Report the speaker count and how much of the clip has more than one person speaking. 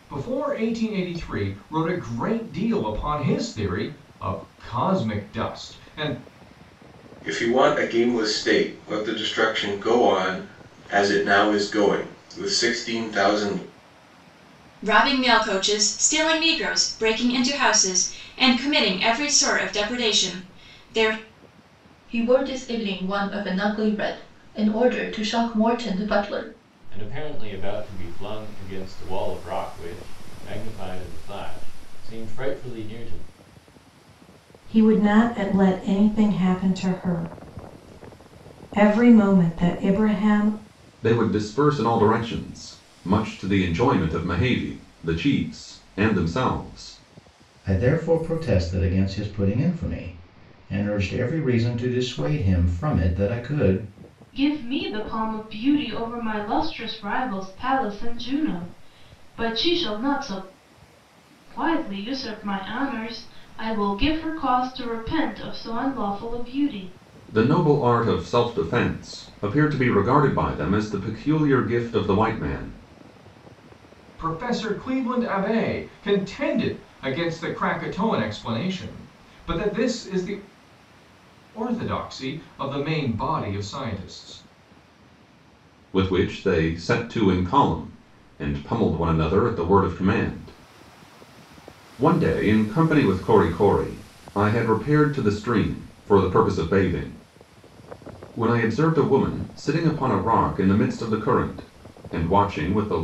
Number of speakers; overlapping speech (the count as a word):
nine, no overlap